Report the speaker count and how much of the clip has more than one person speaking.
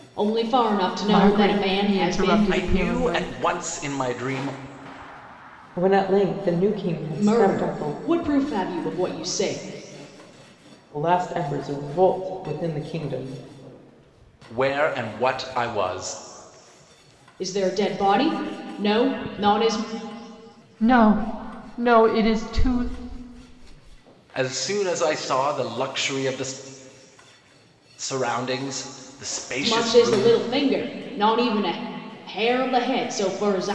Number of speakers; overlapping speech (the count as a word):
four, about 11%